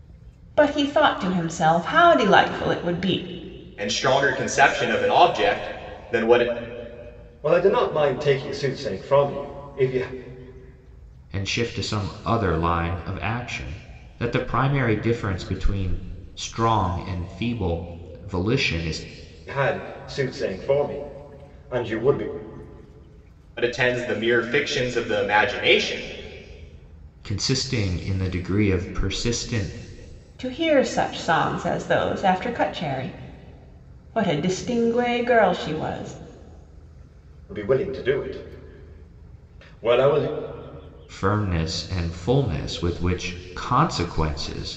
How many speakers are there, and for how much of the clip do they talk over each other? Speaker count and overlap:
four, no overlap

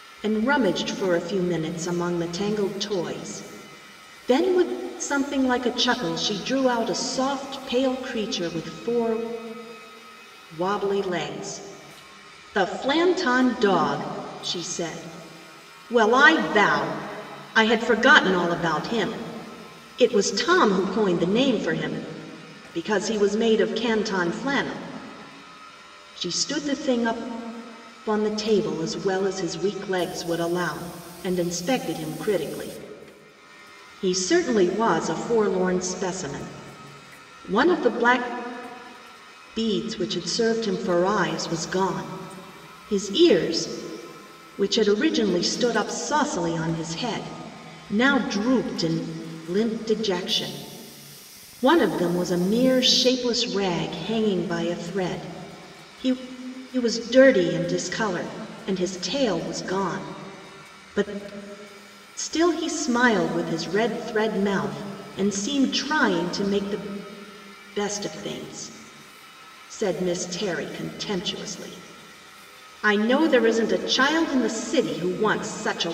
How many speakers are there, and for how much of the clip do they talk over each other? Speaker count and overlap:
one, no overlap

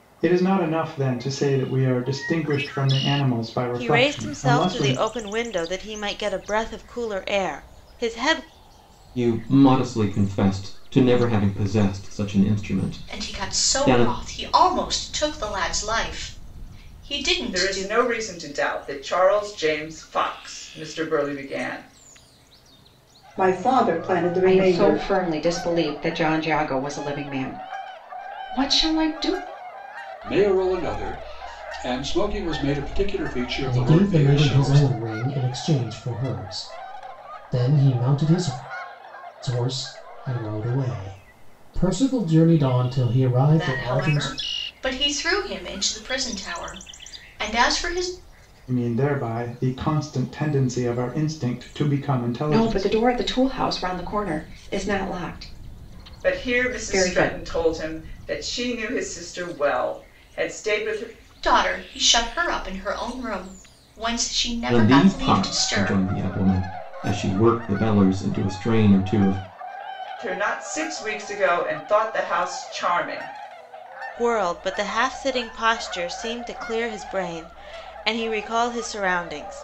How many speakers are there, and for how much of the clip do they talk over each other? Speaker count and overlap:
nine, about 11%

